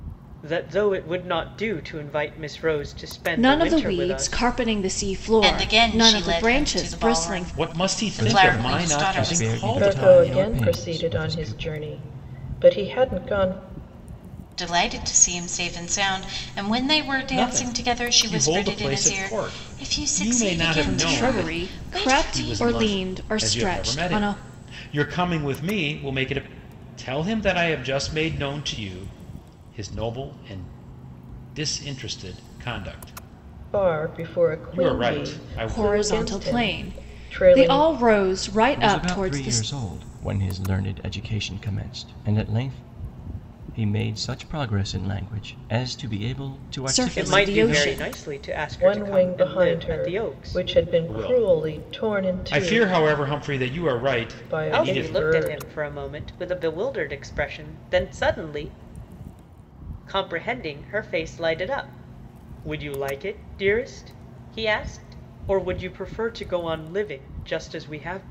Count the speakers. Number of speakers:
6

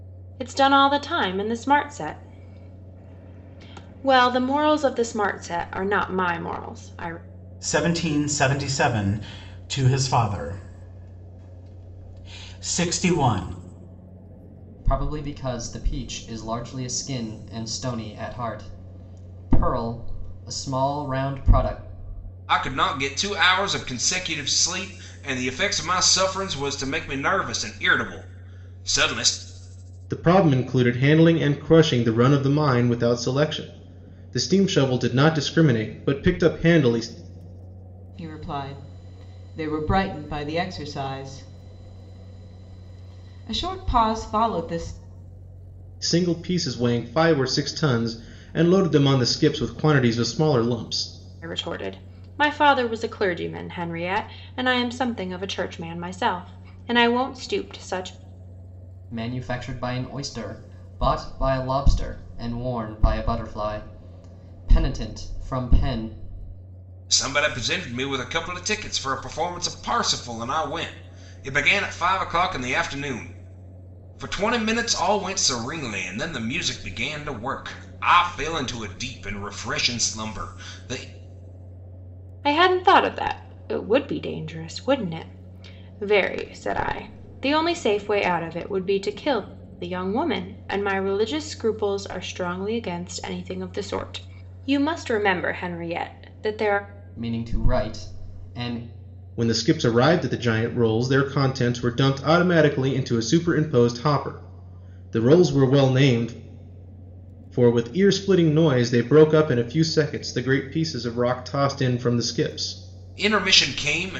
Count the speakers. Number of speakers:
6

